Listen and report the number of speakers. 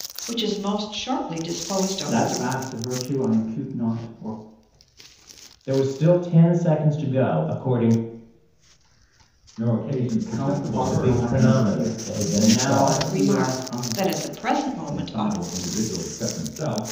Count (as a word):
four